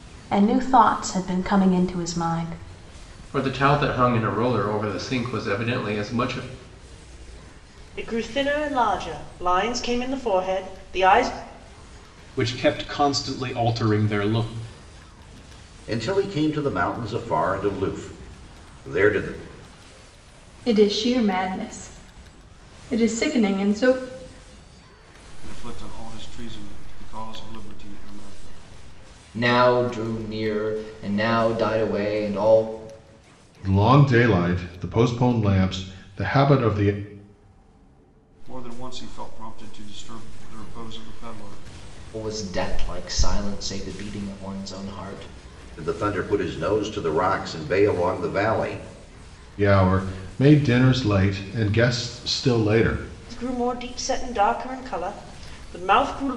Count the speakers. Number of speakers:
9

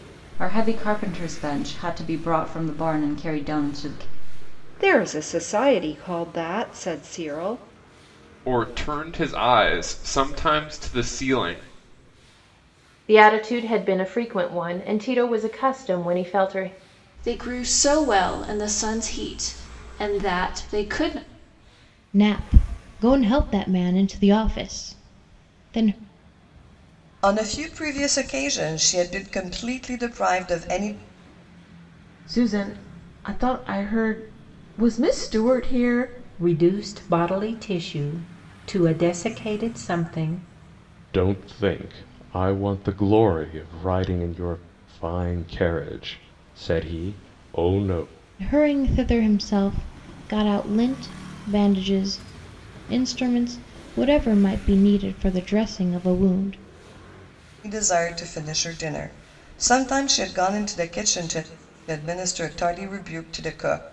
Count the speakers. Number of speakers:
10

